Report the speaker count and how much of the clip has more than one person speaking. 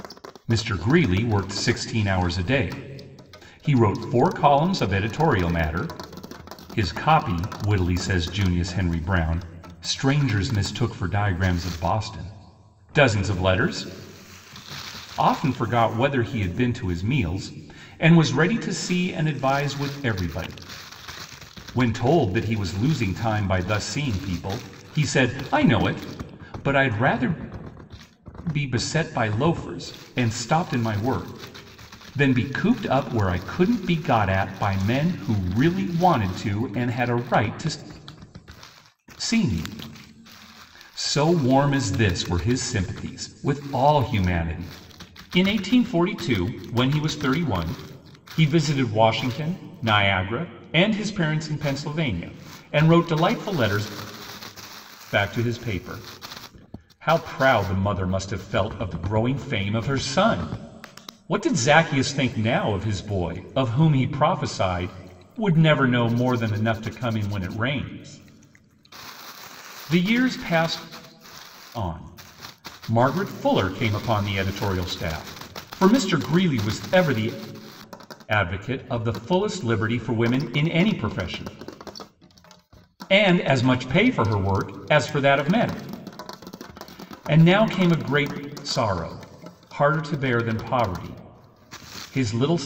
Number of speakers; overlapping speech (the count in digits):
1, no overlap